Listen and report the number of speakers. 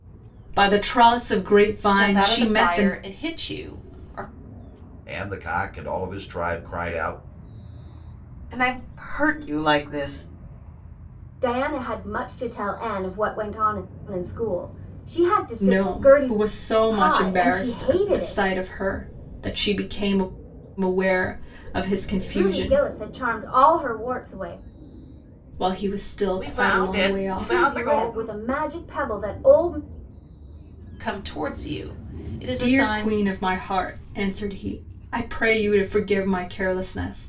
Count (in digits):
5